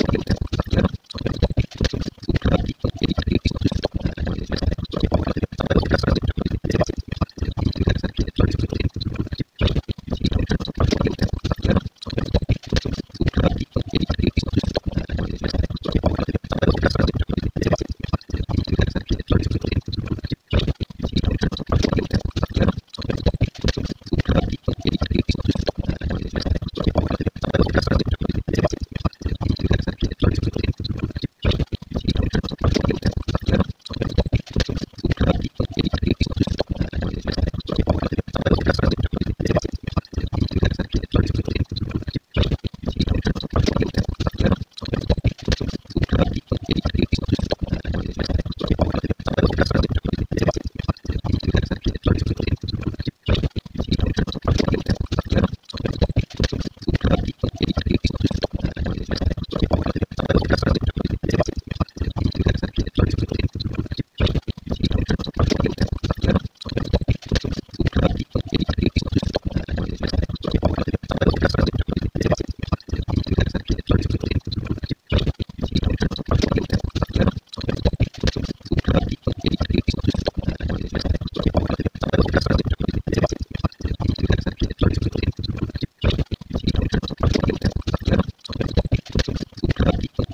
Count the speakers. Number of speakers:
0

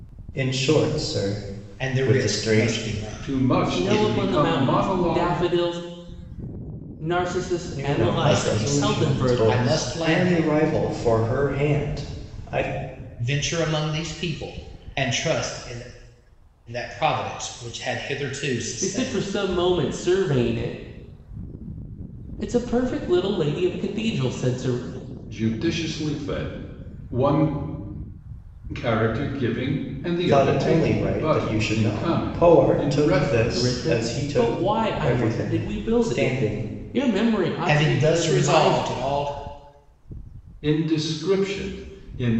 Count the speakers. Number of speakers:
4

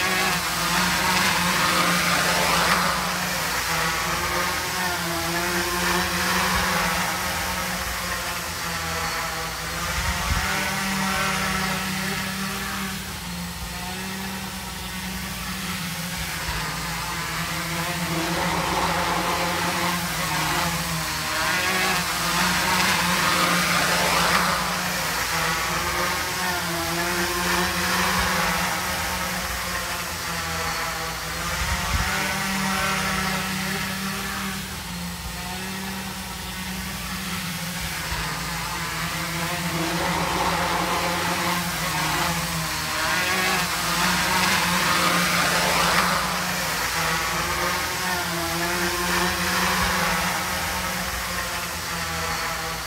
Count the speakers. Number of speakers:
0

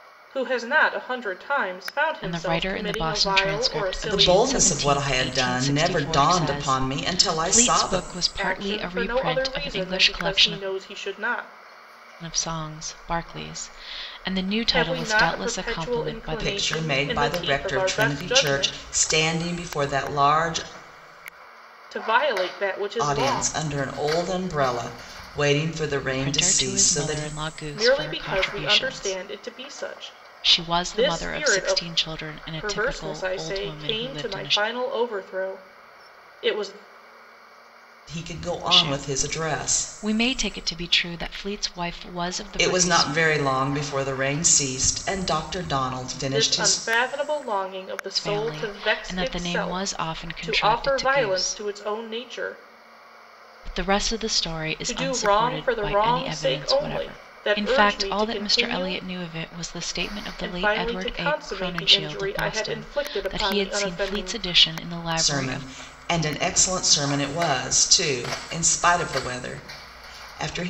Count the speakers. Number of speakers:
3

